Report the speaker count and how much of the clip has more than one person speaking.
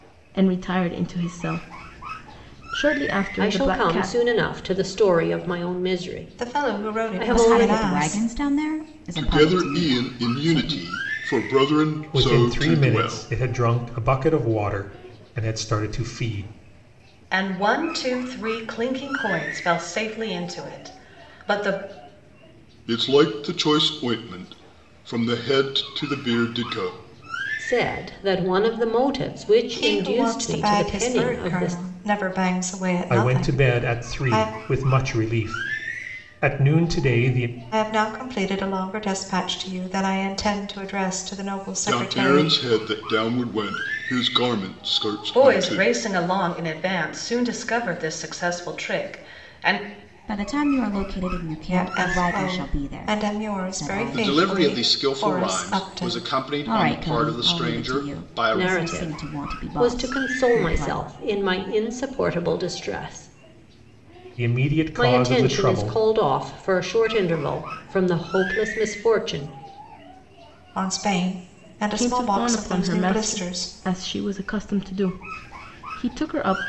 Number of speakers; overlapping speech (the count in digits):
7, about 29%